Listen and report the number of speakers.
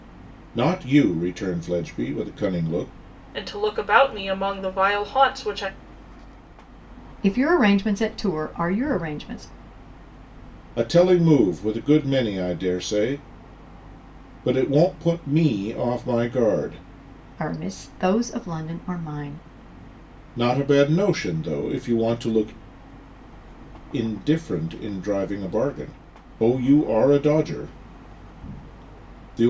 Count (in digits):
3